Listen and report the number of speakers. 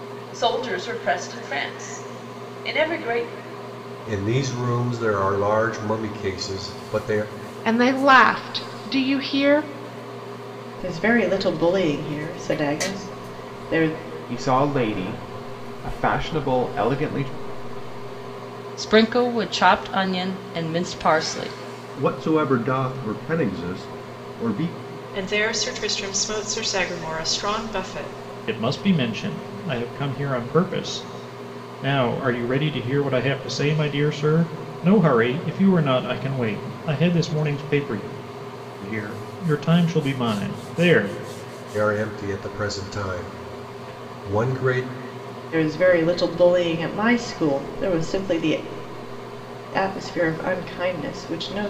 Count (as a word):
nine